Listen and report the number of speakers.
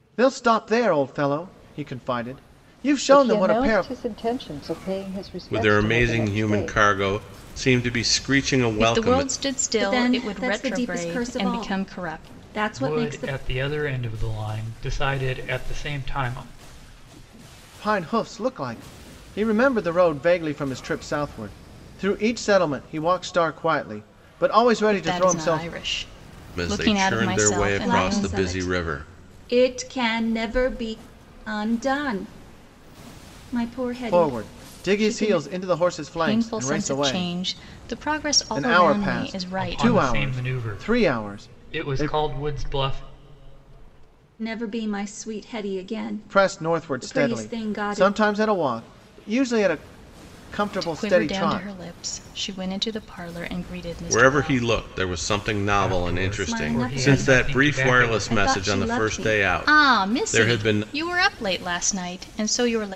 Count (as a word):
six